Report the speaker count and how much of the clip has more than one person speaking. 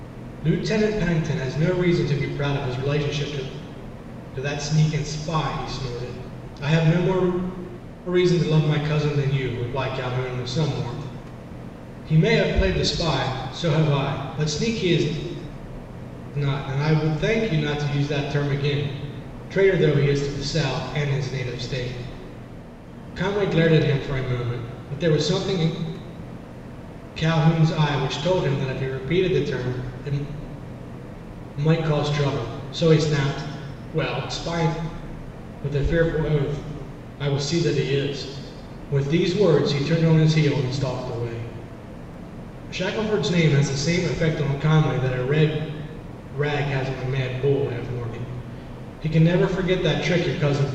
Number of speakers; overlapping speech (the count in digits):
1, no overlap